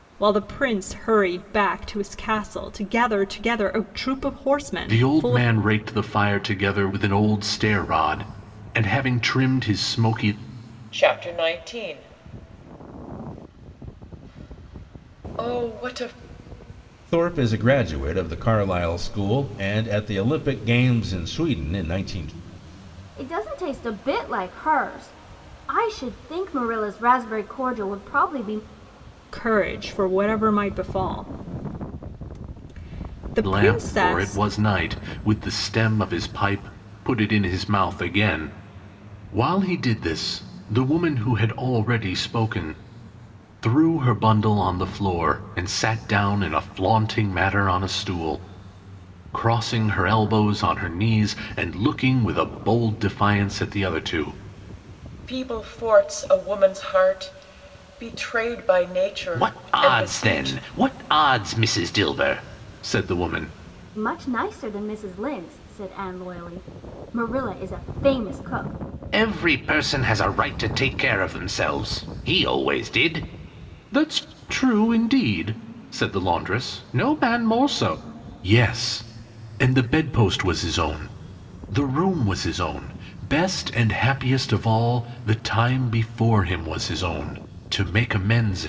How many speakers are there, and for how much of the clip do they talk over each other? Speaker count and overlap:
five, about 3%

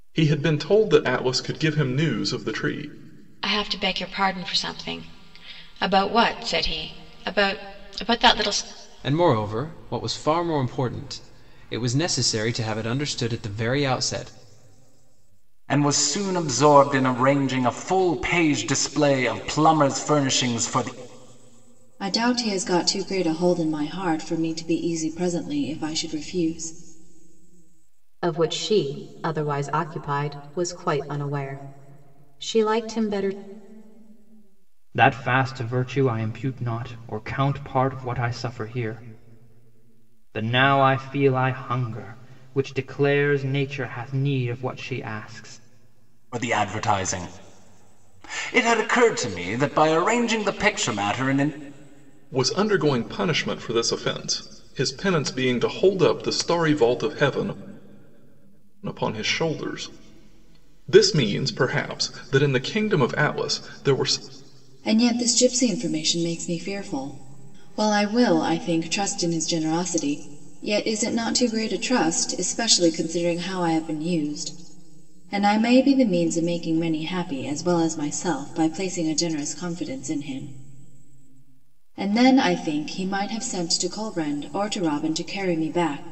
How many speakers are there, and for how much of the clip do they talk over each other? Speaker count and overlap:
seven, no overlap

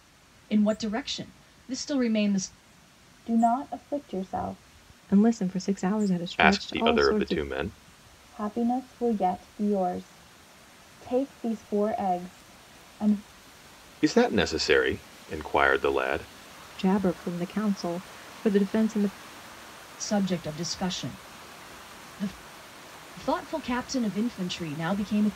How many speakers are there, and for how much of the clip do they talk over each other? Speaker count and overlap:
four, about 4%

